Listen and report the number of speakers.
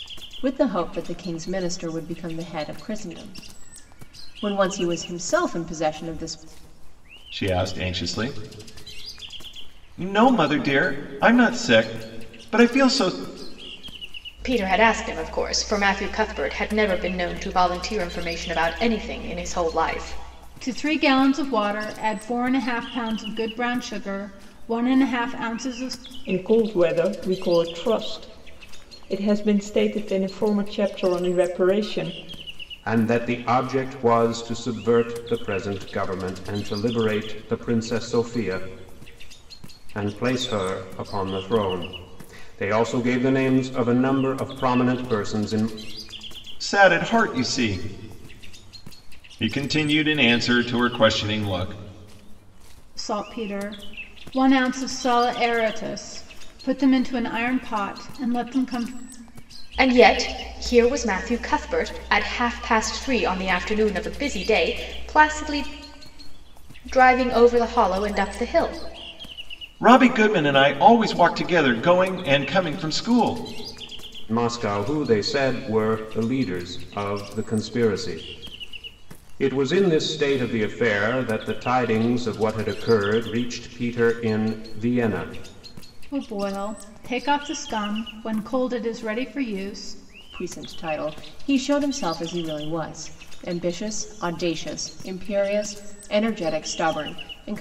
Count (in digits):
6